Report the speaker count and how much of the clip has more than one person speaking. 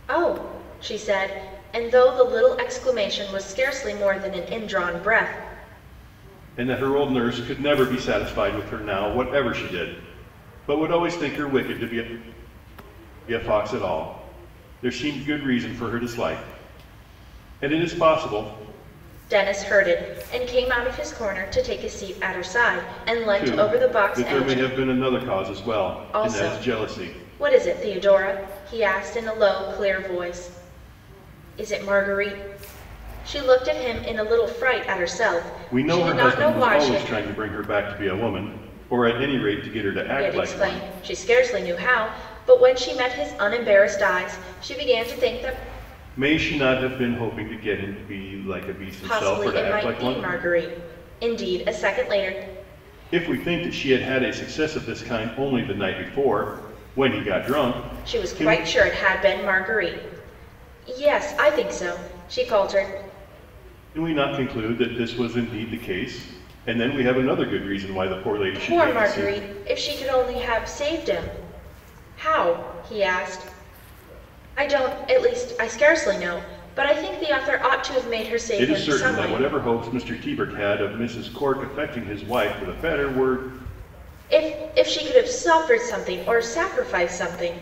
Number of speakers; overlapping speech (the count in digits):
2, about 9%